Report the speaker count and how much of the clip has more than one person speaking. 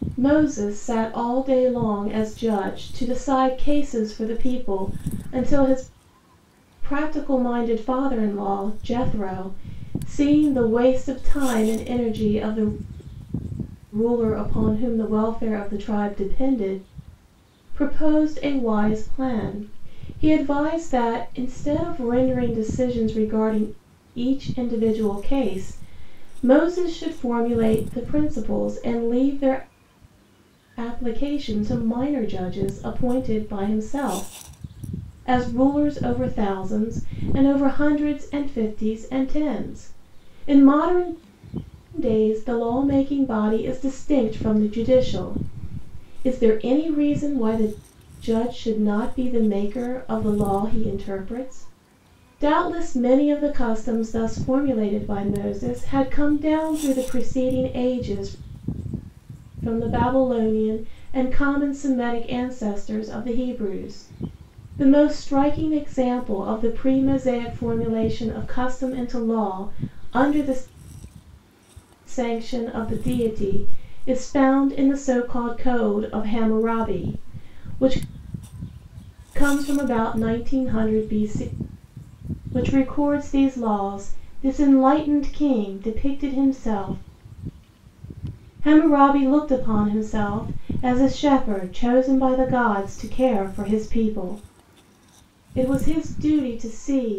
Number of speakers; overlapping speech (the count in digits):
1, no overlap